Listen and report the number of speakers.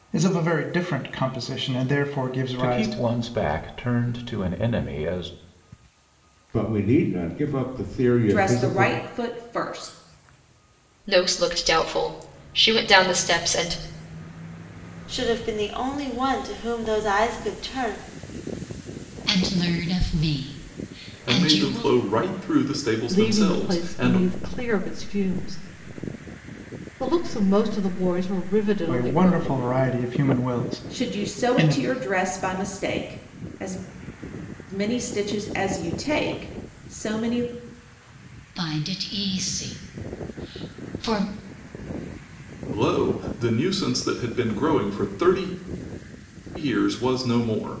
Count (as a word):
nine